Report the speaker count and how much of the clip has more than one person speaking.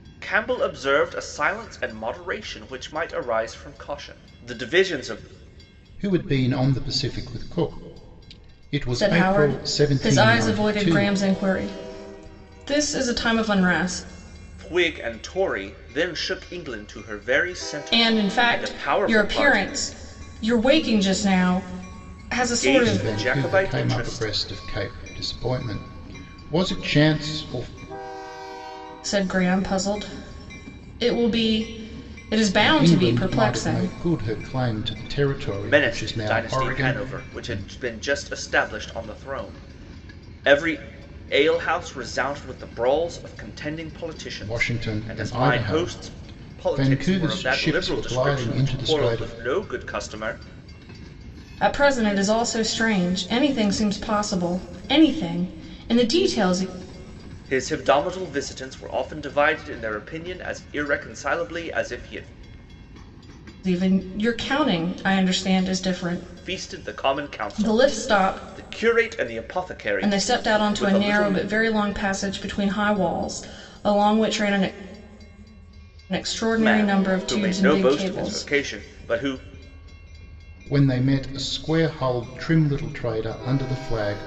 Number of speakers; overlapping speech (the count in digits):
3, about 23%